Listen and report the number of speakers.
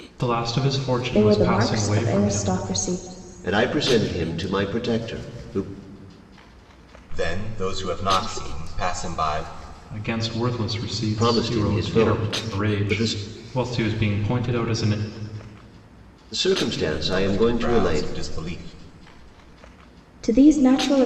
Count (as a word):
four